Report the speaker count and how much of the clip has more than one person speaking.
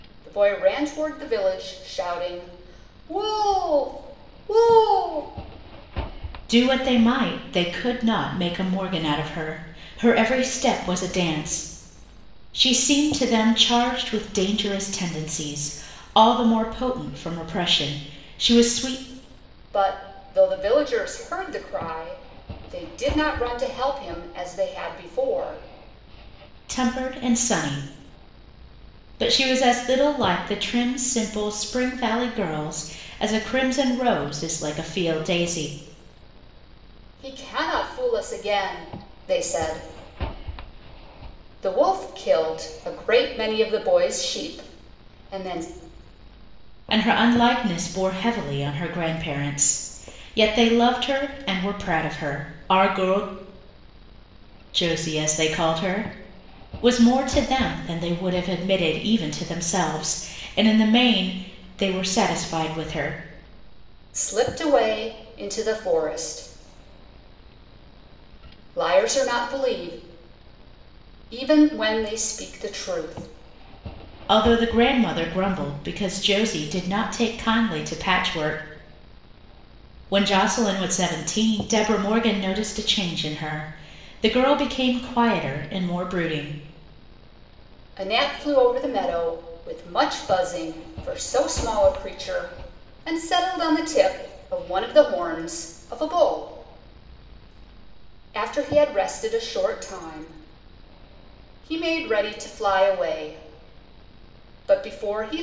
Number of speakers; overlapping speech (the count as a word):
two, no overlap